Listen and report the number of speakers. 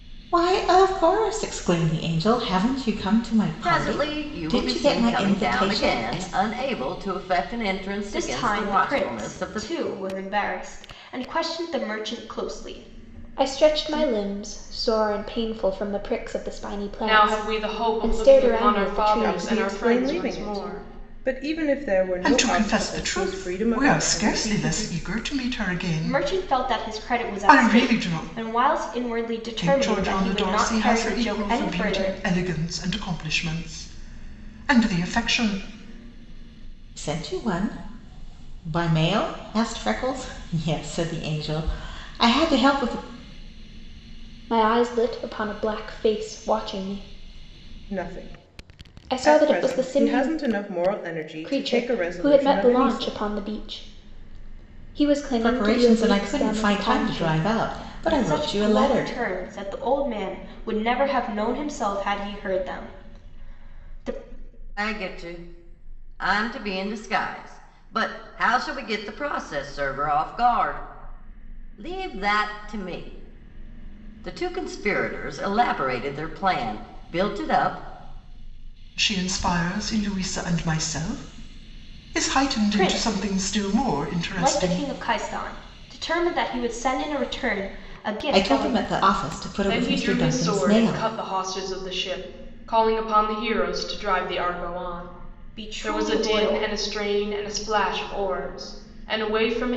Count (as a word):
seven